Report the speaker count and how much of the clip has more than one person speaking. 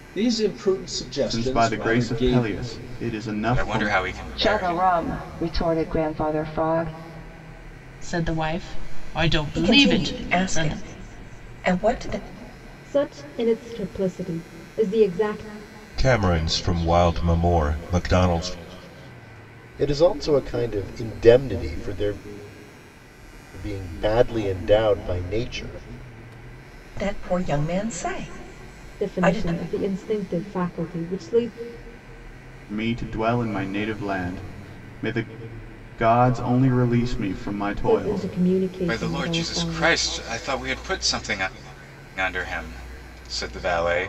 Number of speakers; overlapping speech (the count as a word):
nine, about 14%